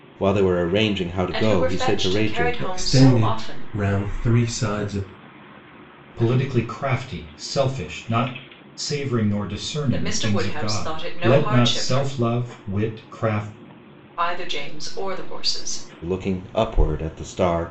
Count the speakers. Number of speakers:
4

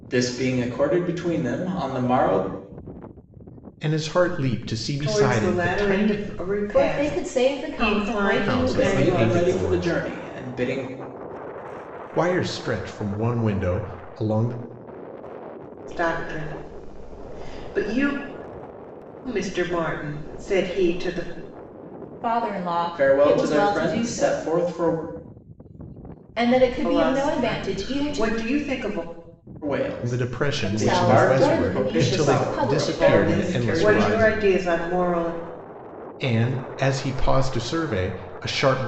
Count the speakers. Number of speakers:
4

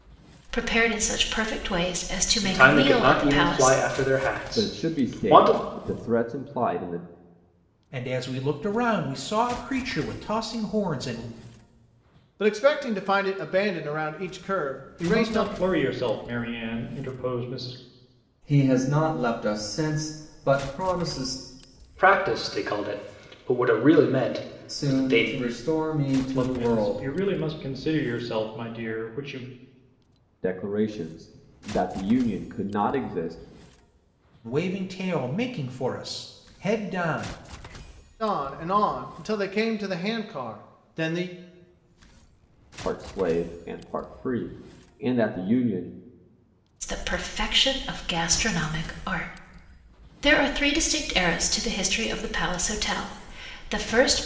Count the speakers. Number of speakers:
7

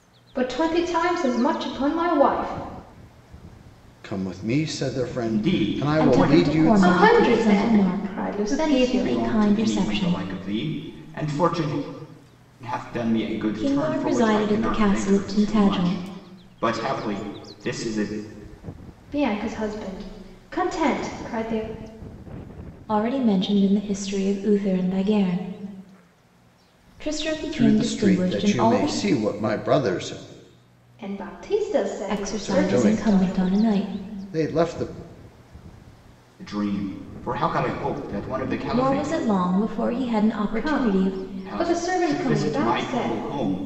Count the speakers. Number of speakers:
4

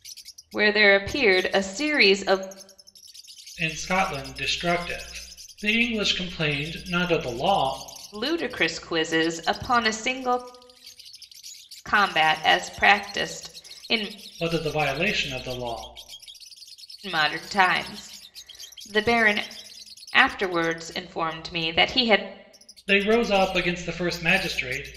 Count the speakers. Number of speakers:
2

